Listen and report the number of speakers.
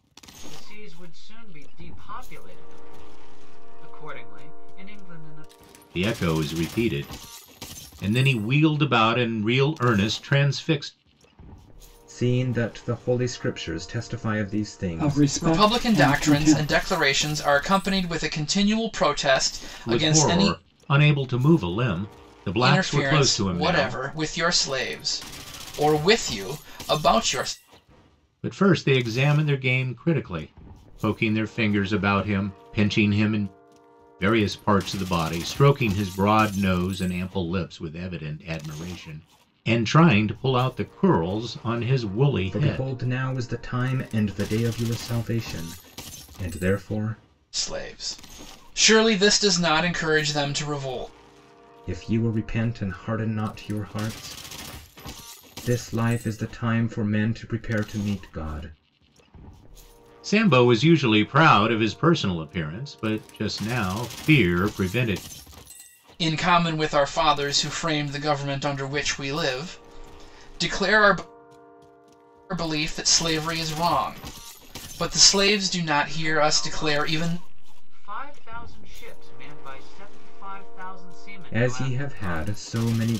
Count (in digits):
5